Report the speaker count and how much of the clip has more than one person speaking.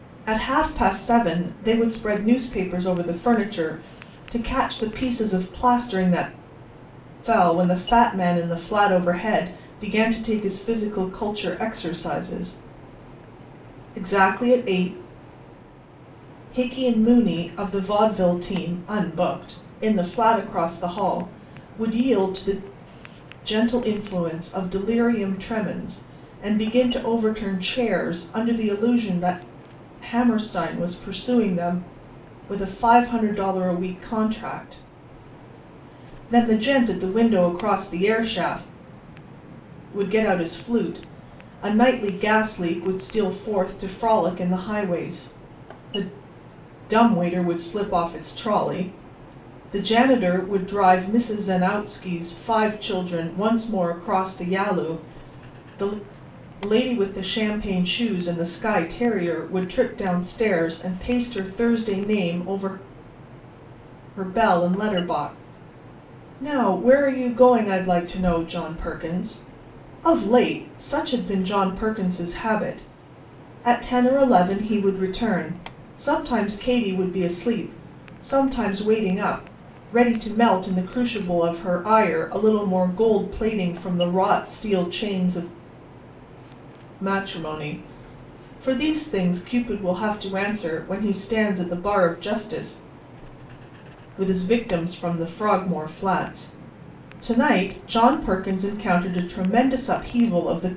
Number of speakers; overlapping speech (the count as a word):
one, no overlap